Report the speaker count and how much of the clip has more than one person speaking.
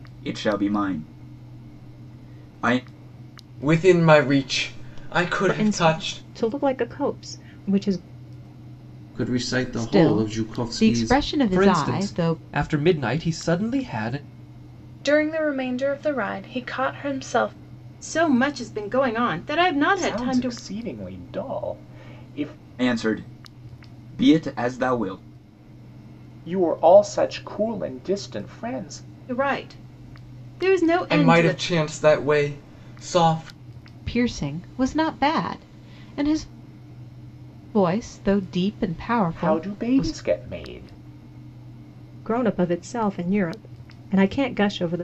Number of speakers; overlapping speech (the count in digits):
9, about 12%